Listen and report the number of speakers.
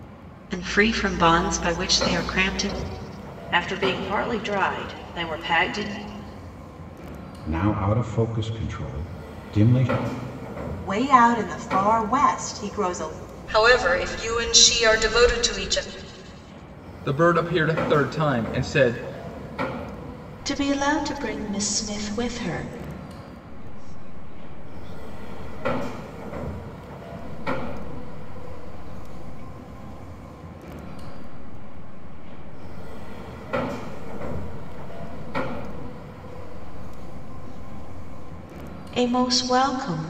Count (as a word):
eight